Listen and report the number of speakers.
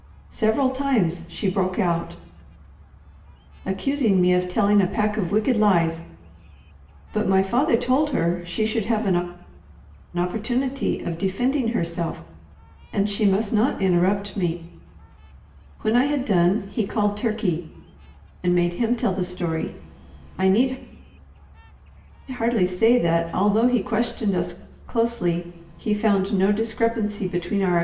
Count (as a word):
one